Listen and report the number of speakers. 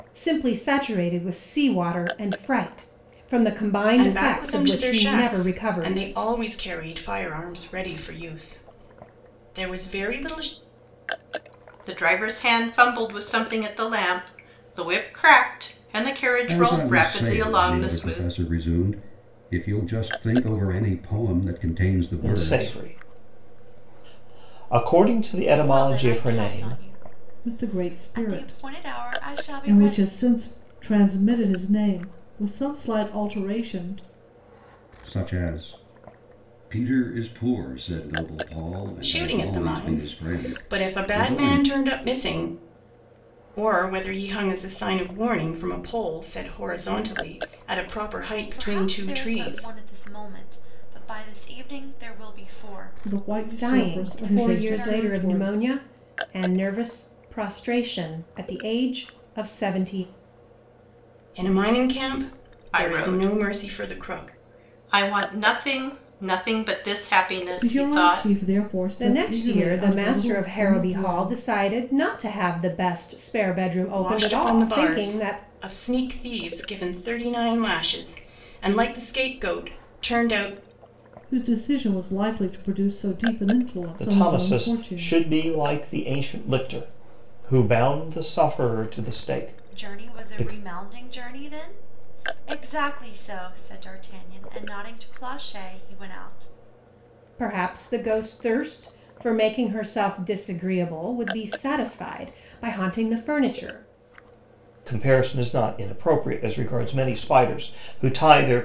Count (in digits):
7